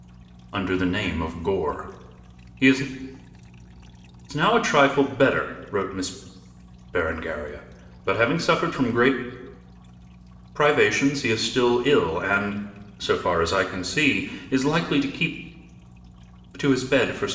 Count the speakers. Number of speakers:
one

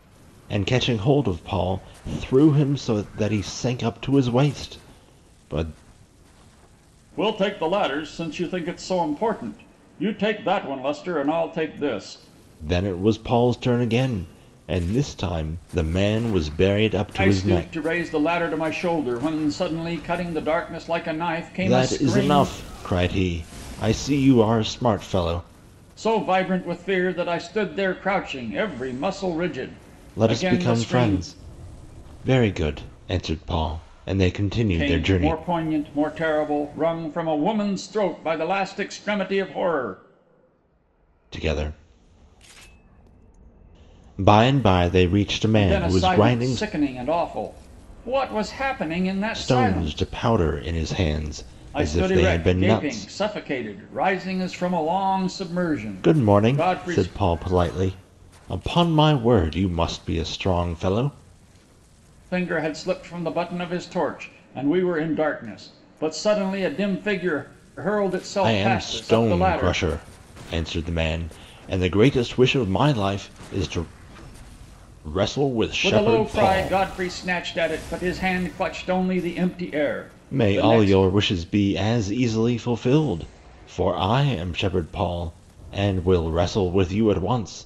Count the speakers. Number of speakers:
two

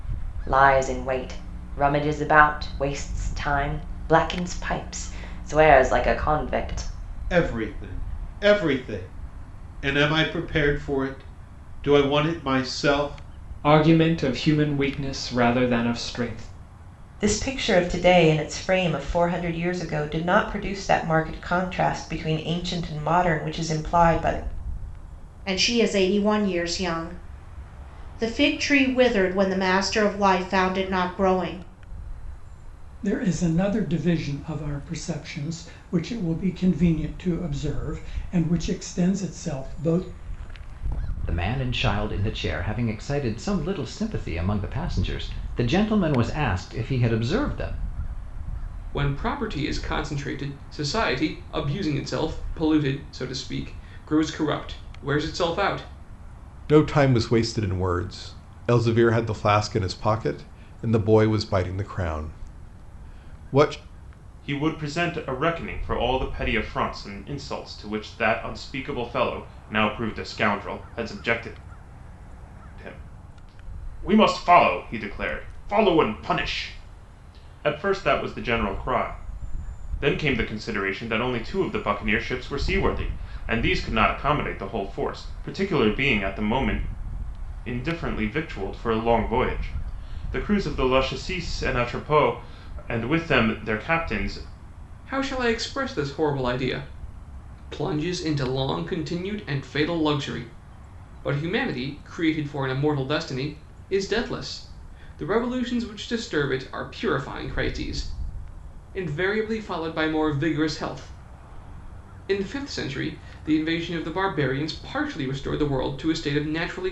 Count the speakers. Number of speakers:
ten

